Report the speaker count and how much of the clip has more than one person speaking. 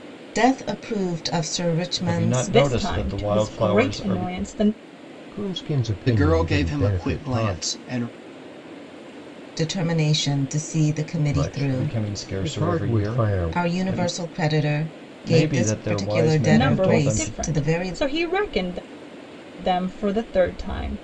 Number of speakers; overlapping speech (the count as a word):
five, about 45%